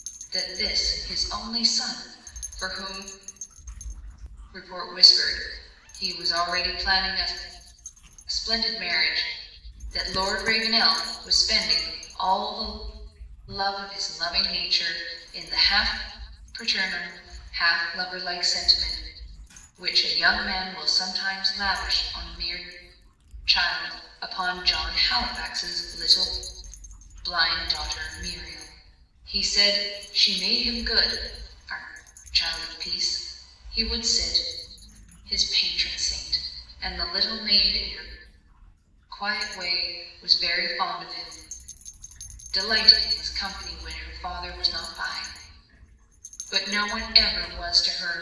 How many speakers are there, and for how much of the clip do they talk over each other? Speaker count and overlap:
1, no overlap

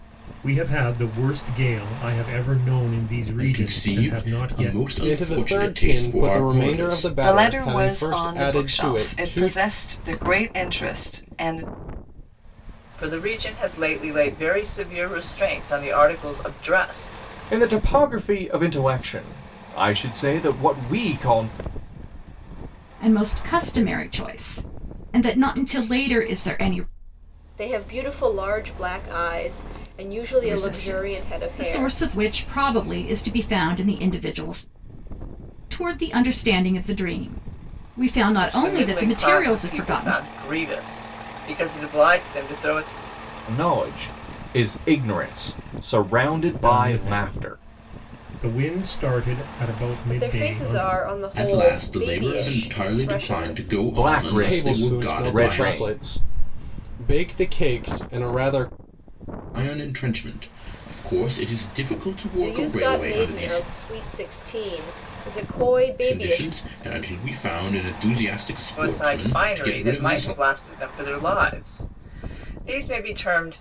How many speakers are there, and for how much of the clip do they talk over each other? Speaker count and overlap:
8, about 26%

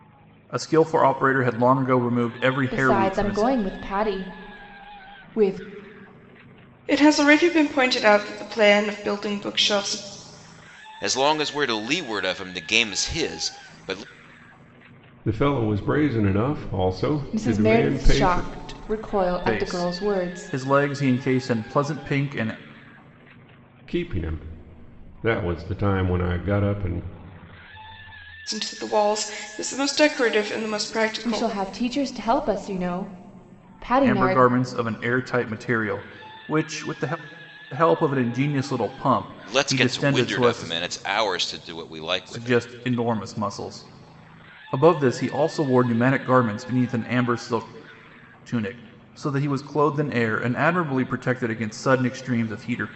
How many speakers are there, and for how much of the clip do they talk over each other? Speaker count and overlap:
5, about 11%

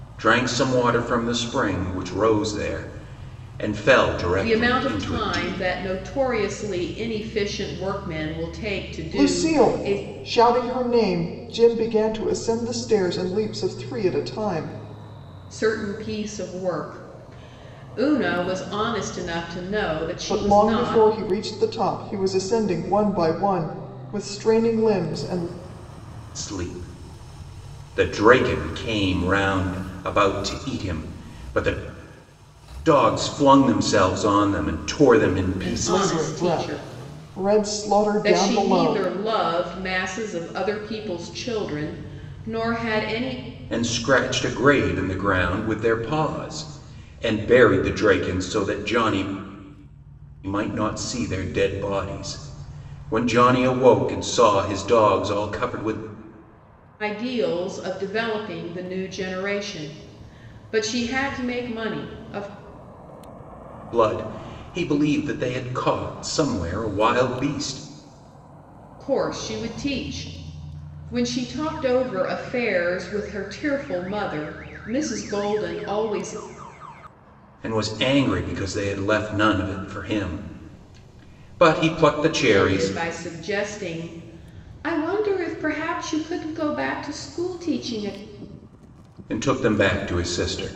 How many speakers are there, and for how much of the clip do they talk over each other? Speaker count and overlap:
3, about 6%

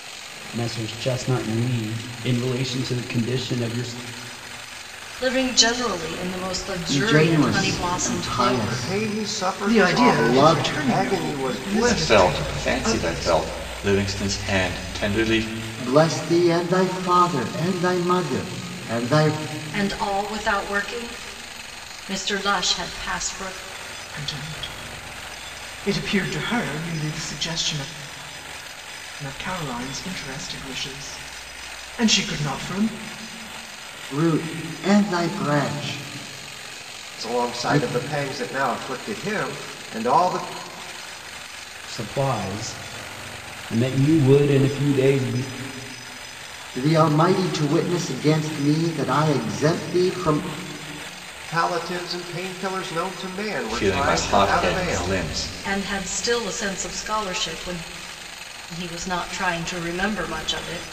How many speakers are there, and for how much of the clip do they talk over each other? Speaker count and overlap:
6, about 15%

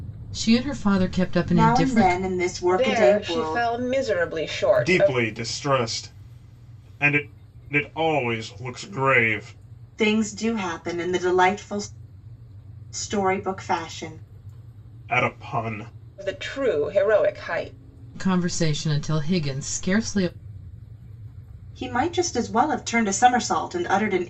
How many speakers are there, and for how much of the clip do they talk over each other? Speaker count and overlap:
4, about 9%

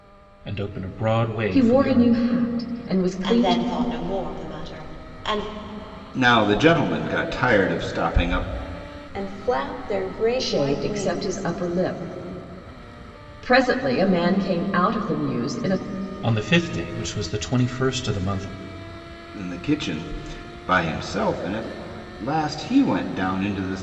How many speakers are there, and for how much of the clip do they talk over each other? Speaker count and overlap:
5, about 9%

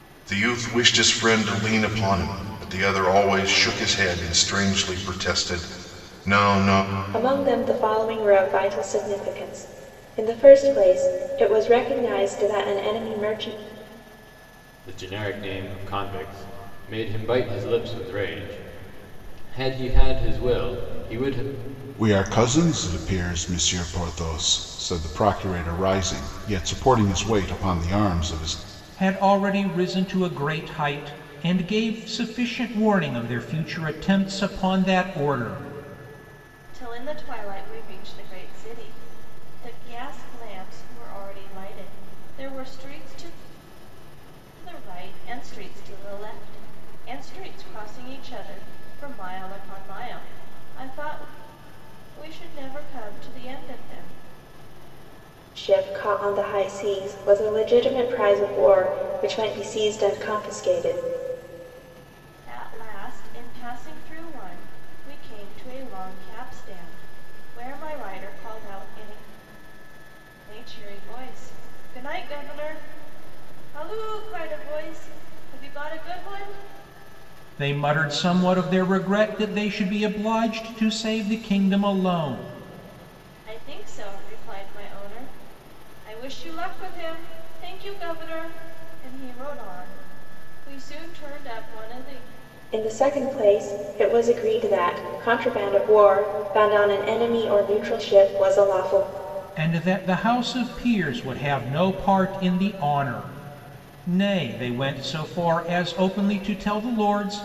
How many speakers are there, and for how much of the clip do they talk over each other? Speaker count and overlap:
6, no overlap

